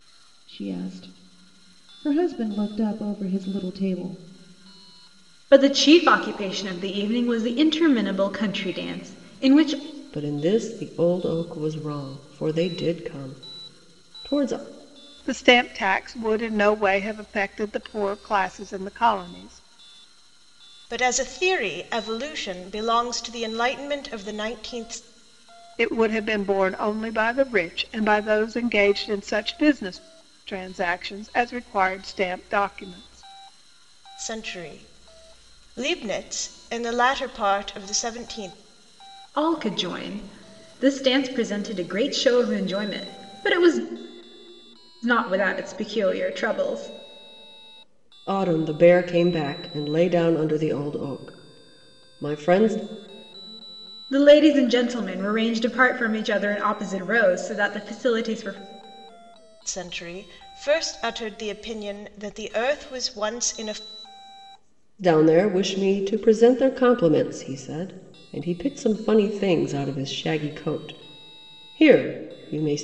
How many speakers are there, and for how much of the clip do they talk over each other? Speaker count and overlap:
five, no overlap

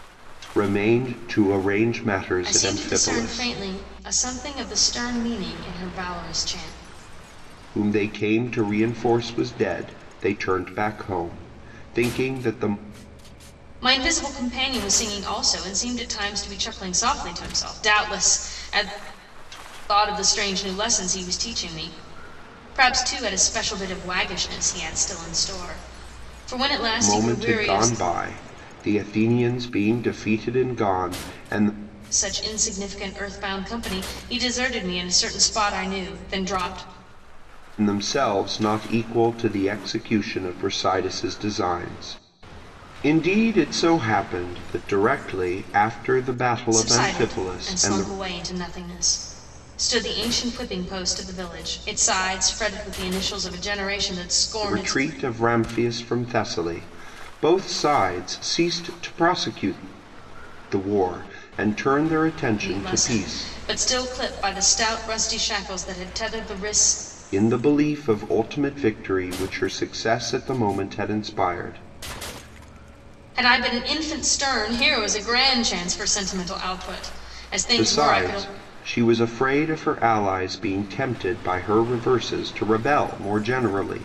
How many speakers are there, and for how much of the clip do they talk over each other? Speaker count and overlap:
two, about 7%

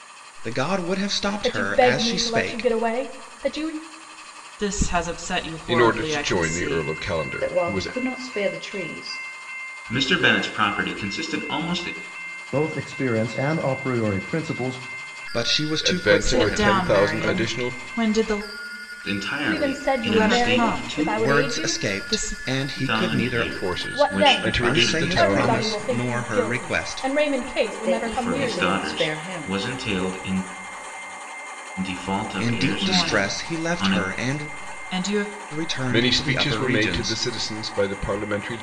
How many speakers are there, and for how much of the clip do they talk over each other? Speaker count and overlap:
seven, about 46%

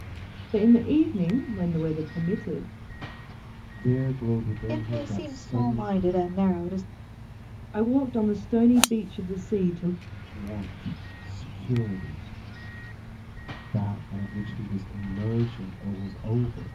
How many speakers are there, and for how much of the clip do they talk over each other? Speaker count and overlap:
three, about 7%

